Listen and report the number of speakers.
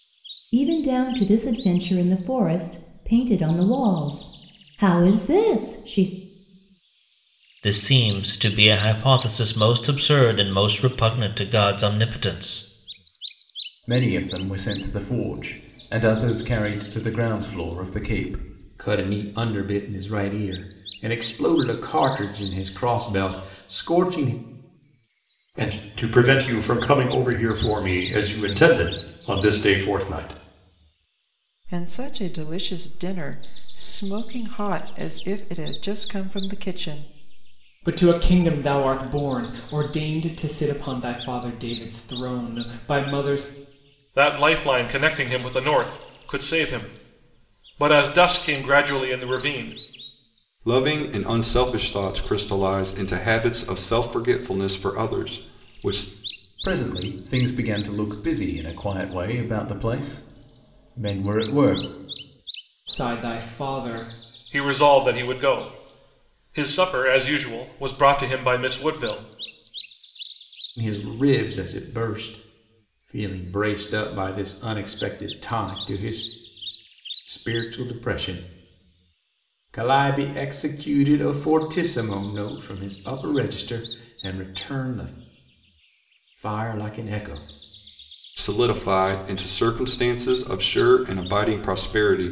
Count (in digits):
9